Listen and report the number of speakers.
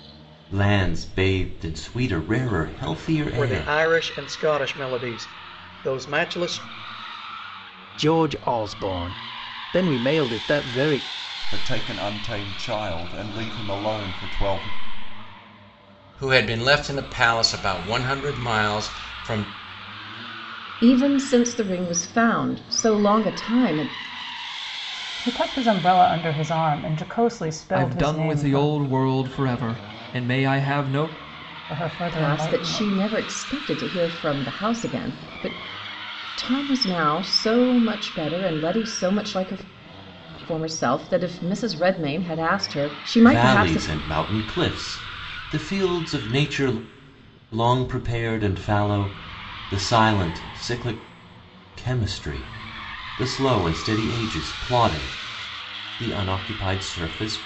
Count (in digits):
8